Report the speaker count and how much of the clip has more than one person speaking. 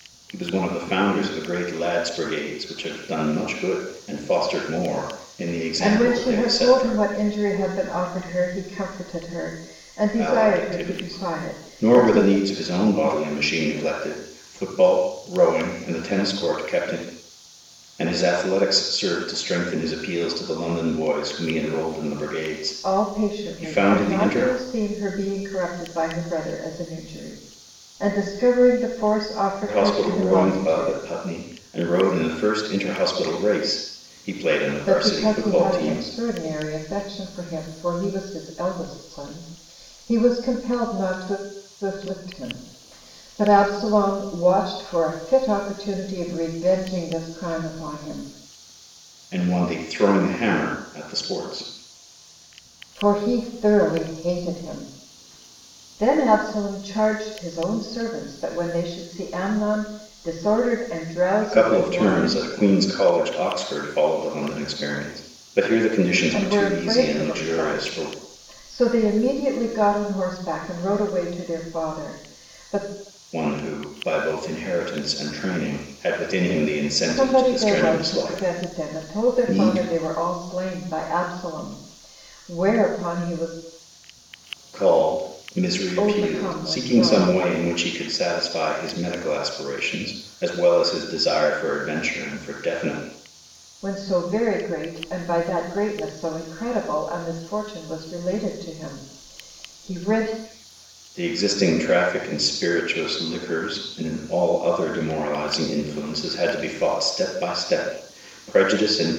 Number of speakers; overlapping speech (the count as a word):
two, about 14%